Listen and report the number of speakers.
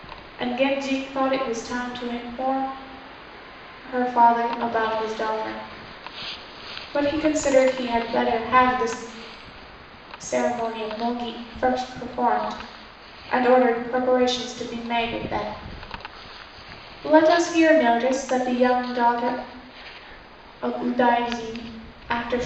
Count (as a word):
one